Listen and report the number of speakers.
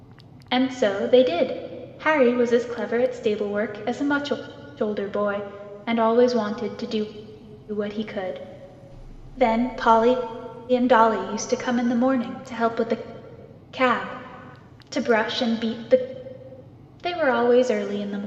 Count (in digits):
1